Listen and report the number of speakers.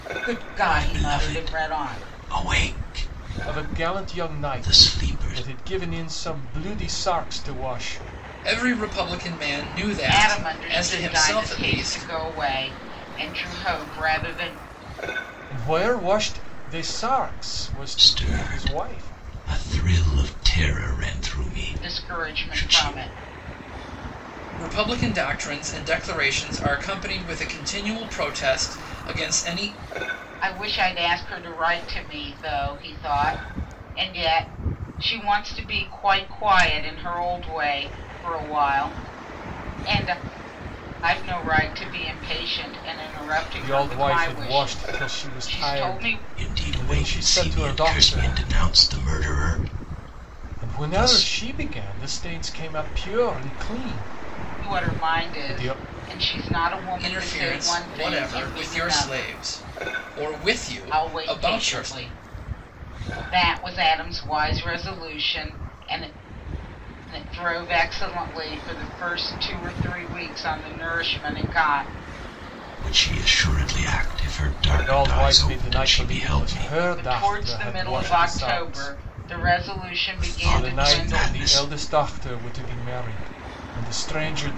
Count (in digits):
4